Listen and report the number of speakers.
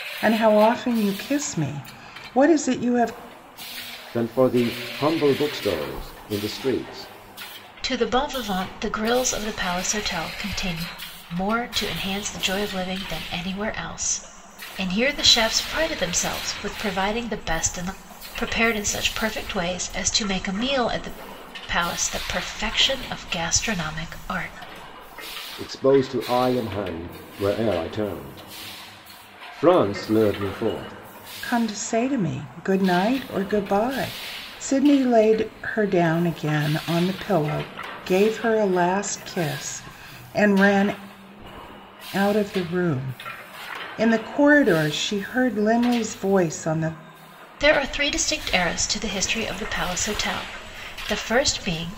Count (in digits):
3